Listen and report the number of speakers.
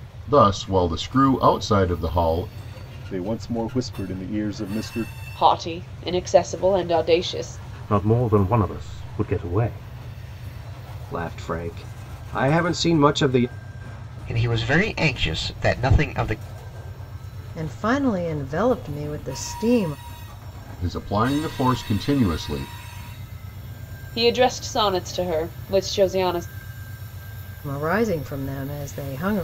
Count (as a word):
seven